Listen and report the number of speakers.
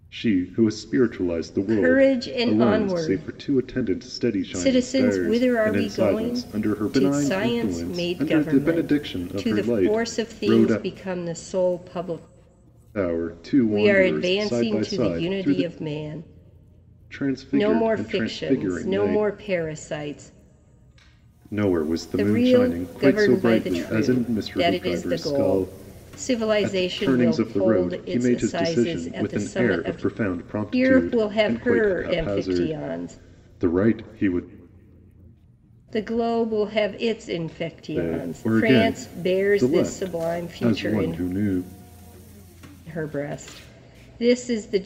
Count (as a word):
two